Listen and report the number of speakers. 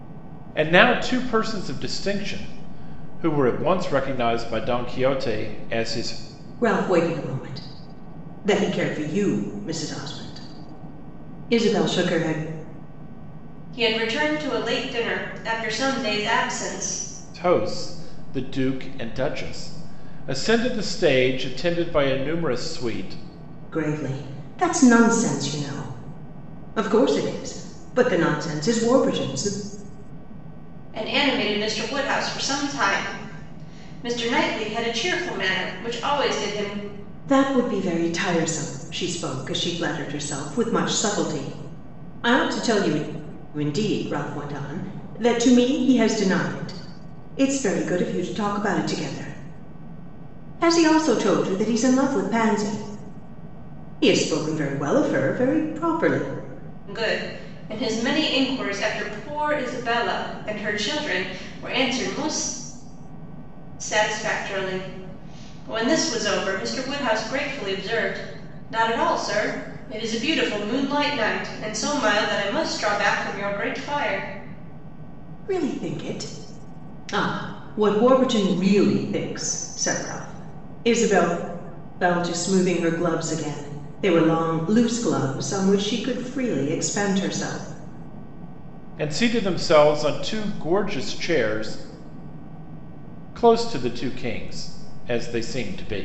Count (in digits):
3